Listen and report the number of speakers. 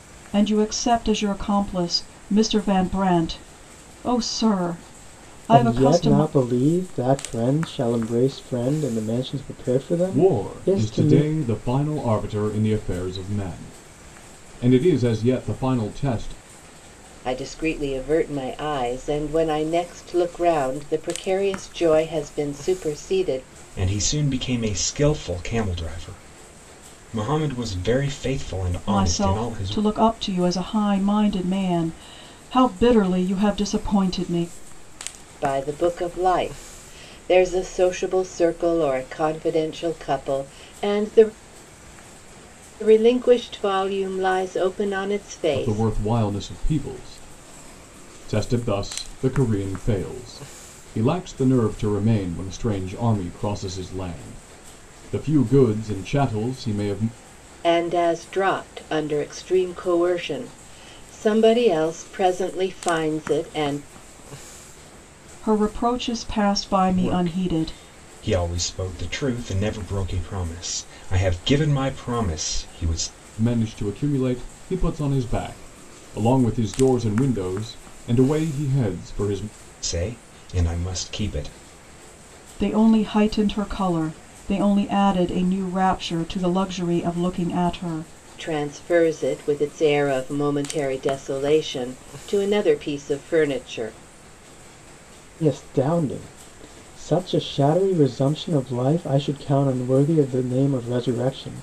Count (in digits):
5